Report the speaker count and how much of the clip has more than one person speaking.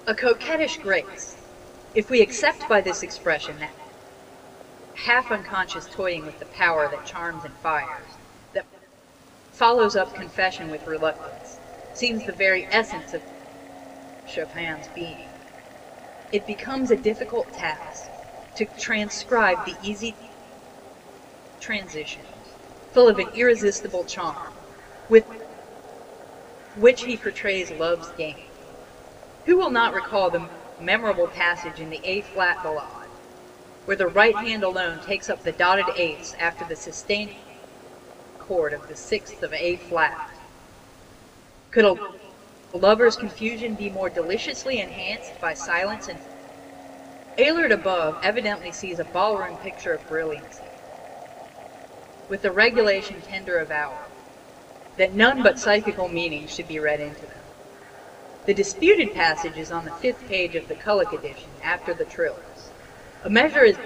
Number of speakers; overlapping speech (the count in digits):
1, no overlap